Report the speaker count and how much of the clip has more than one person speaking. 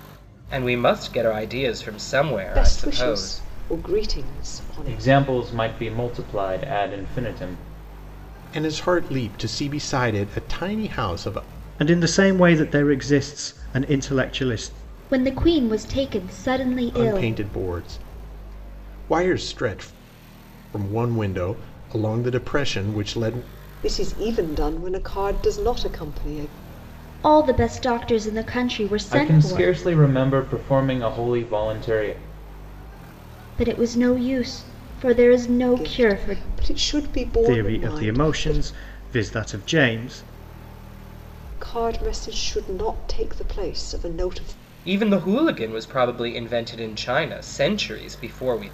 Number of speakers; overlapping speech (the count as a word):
six, about 9%